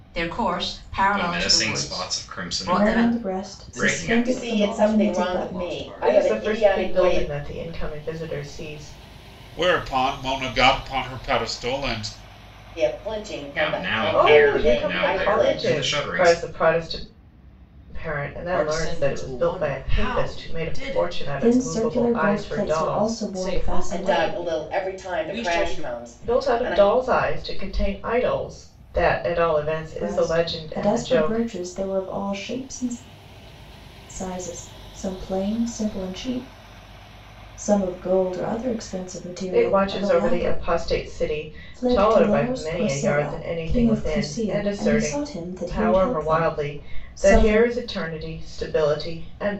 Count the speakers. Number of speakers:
seven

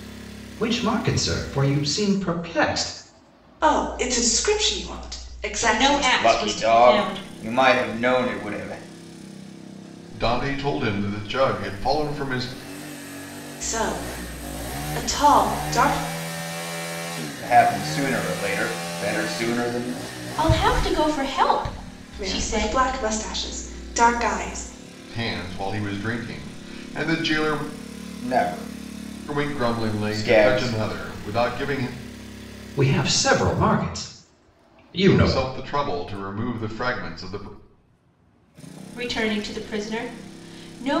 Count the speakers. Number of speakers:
five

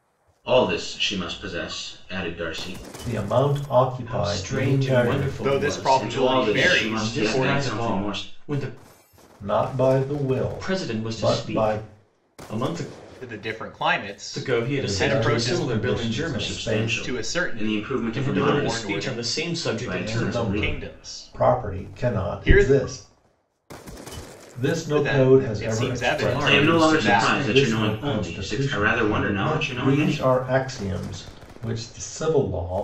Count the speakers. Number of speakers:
four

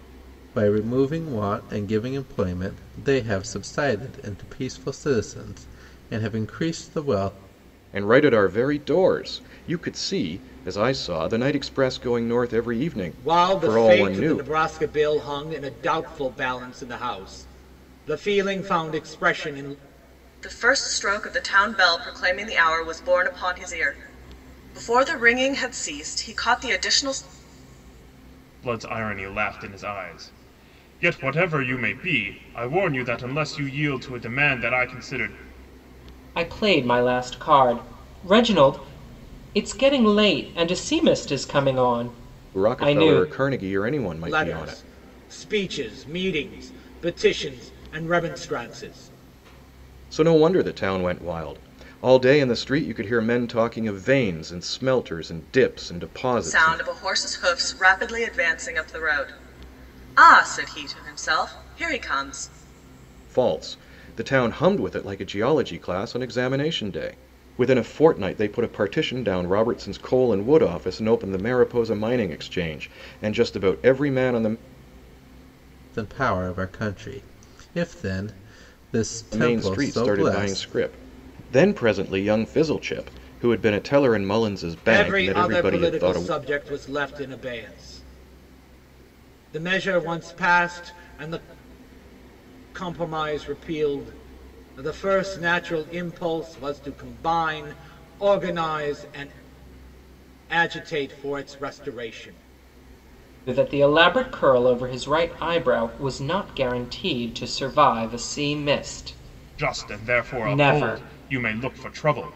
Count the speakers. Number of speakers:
six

